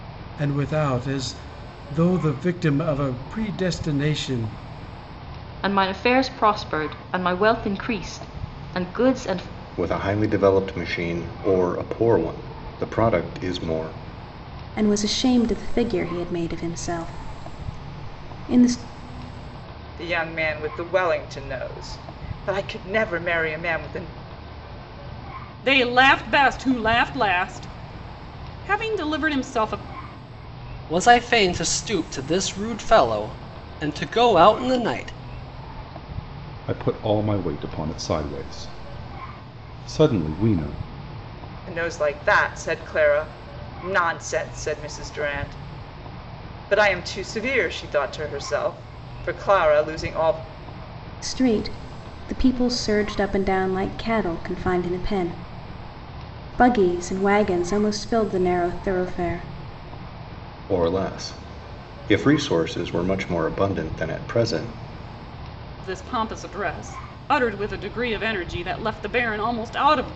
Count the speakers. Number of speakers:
eight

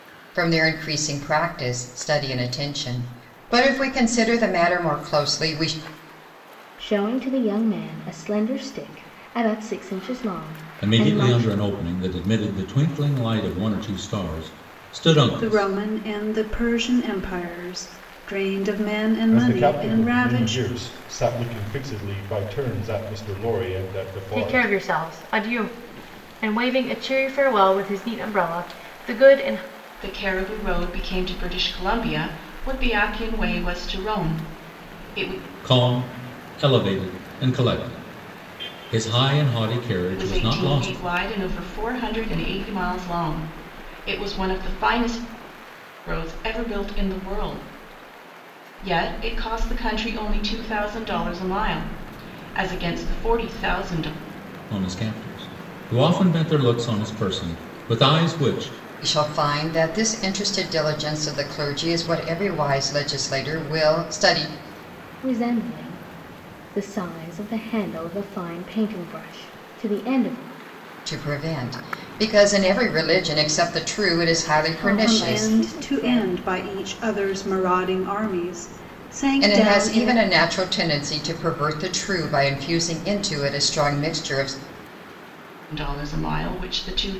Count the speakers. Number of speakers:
seven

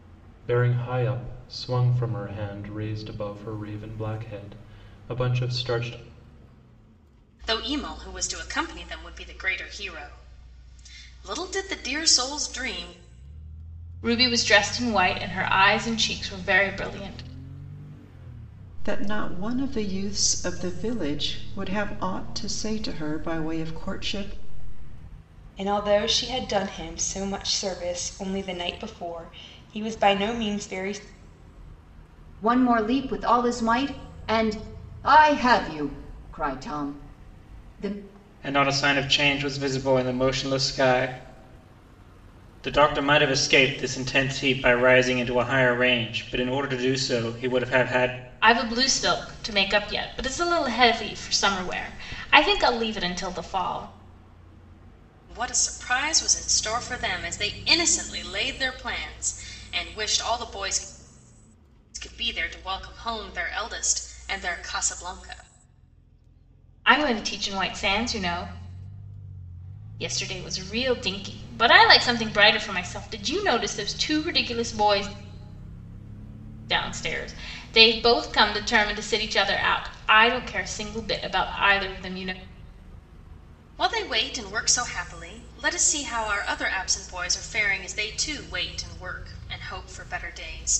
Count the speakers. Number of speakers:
seven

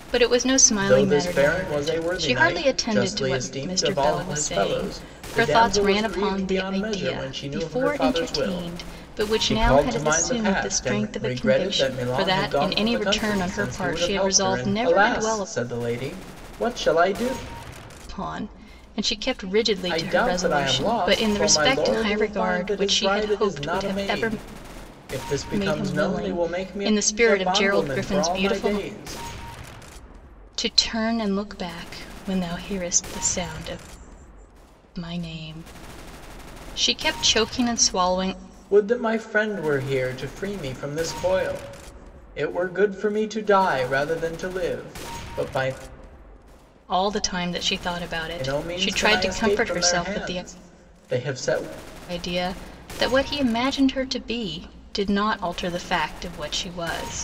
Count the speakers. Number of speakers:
two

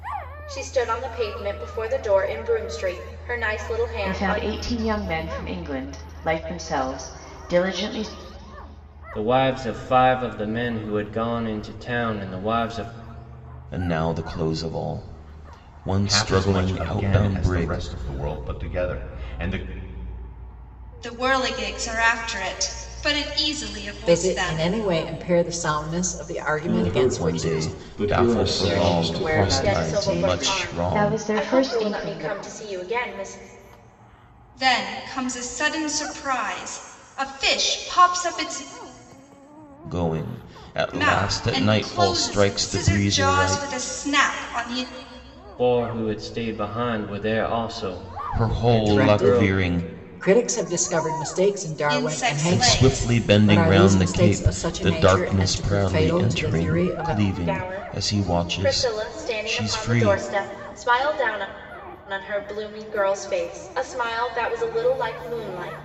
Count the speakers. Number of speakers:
eight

